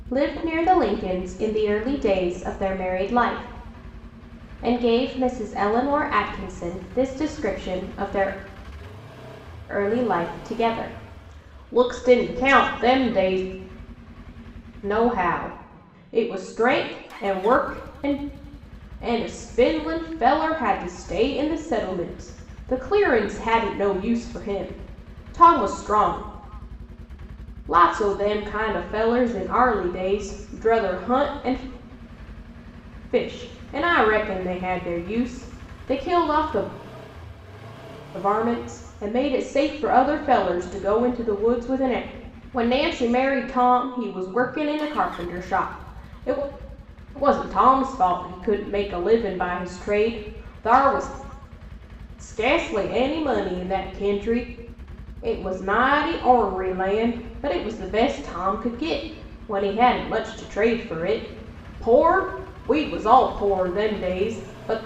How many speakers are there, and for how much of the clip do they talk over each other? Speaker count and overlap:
1, no overlap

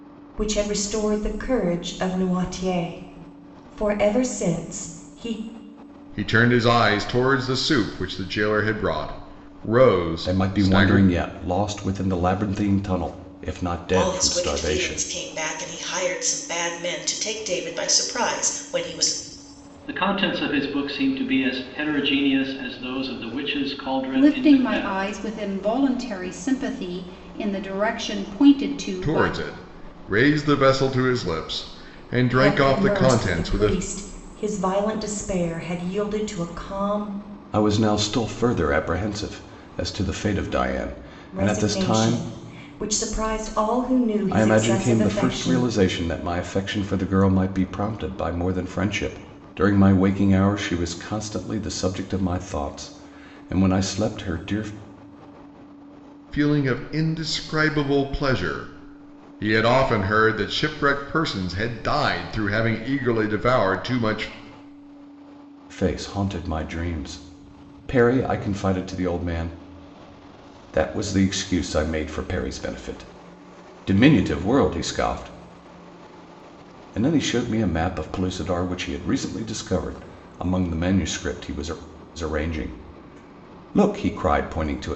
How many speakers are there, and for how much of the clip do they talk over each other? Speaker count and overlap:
6, about 9%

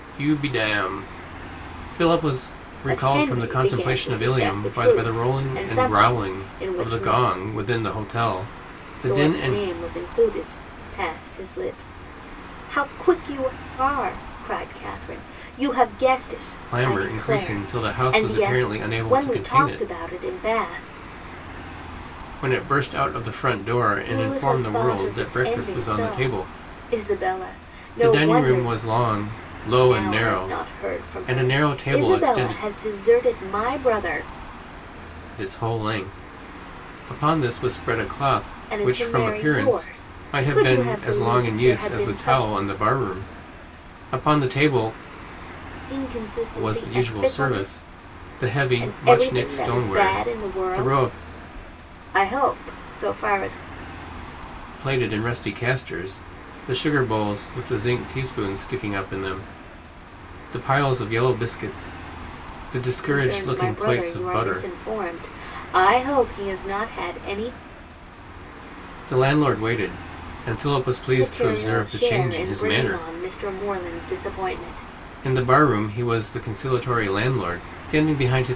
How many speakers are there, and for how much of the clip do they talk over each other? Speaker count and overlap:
2, about 32%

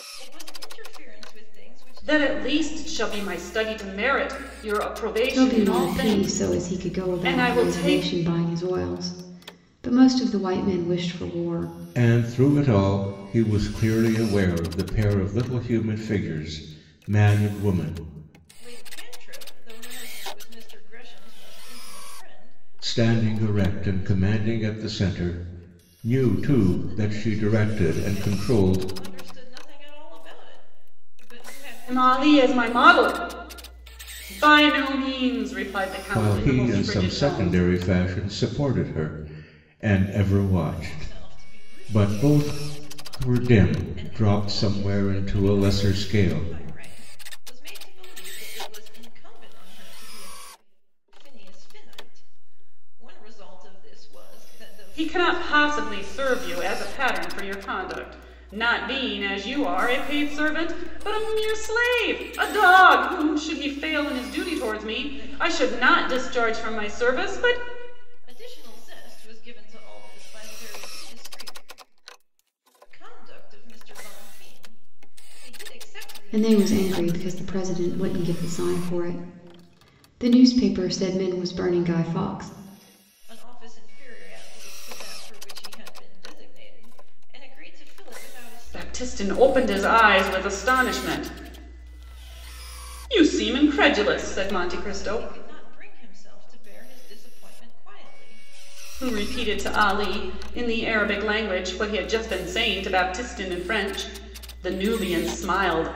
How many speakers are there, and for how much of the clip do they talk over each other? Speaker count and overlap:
4, about 29%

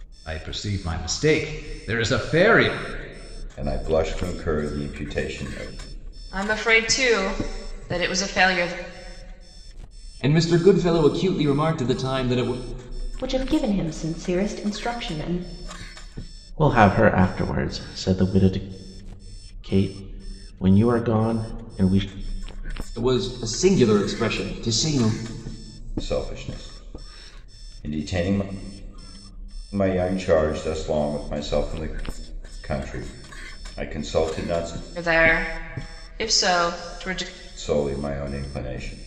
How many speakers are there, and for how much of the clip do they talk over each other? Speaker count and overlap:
6, no overlap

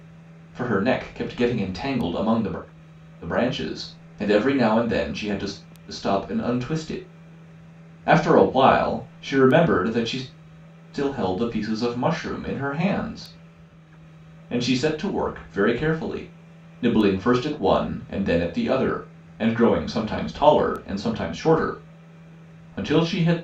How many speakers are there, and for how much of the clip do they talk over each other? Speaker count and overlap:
1, no overlap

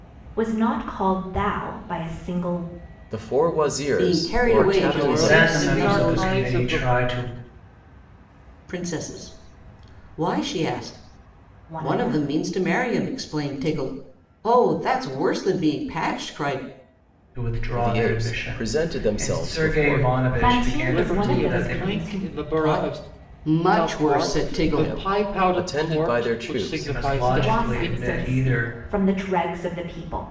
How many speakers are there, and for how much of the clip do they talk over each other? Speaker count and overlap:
5, about 44%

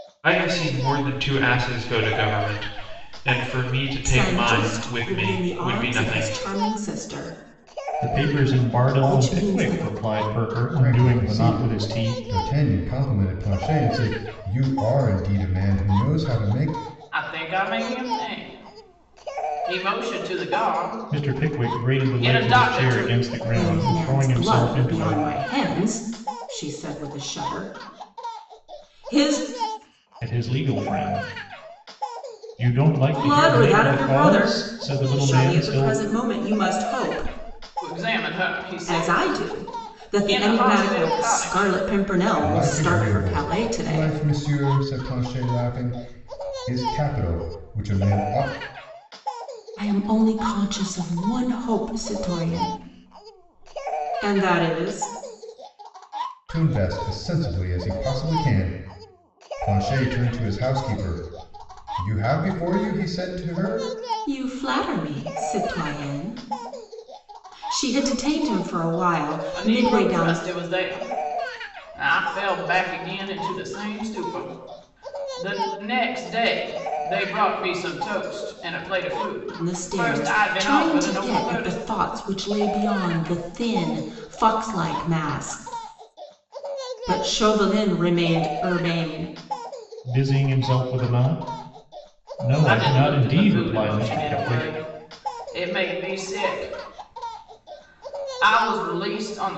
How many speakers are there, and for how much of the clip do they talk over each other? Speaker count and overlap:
5, about 23%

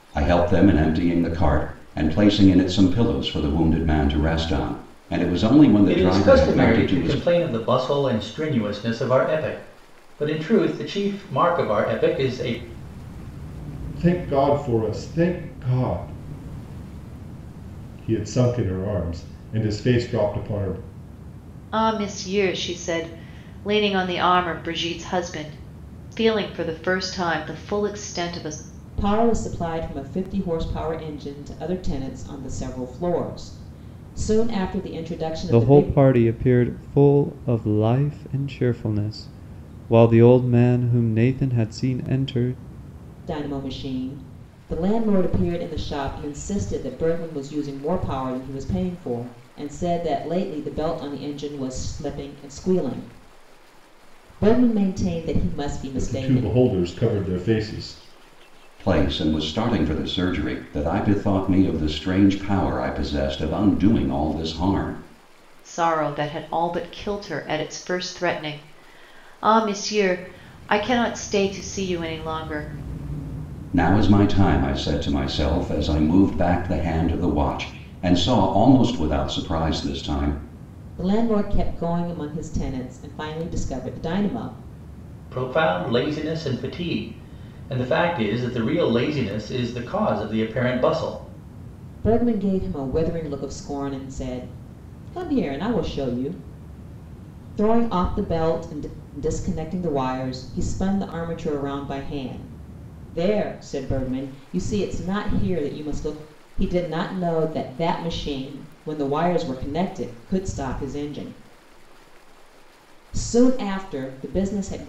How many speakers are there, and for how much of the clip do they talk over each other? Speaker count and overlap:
6, about 2%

